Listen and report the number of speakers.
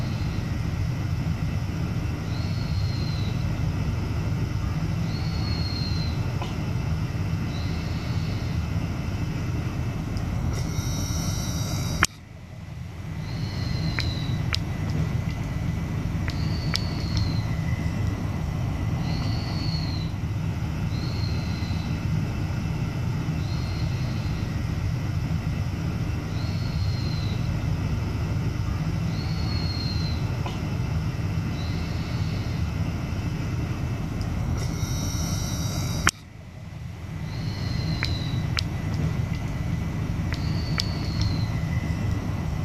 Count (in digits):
0